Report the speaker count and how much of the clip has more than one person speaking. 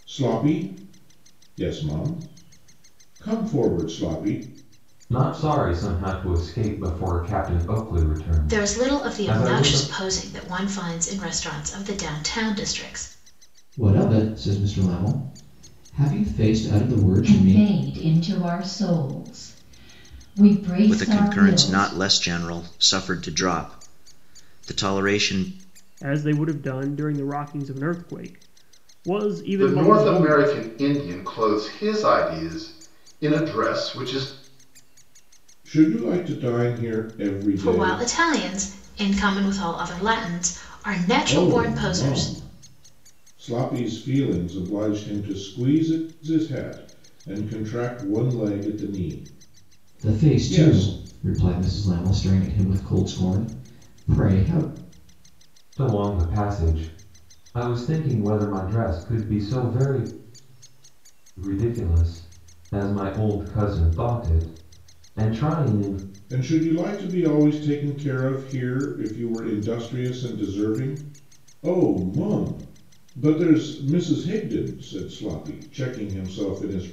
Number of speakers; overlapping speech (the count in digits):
8, about 9%